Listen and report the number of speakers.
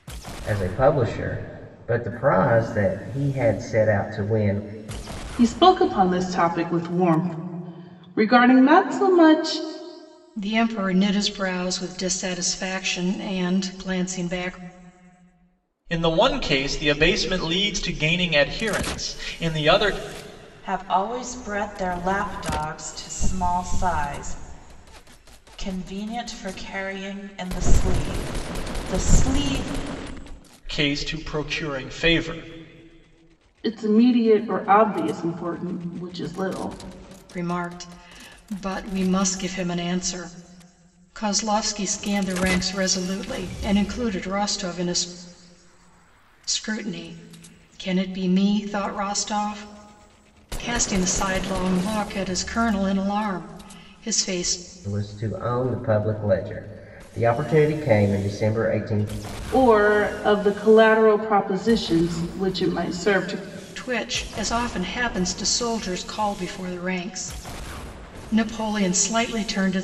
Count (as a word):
five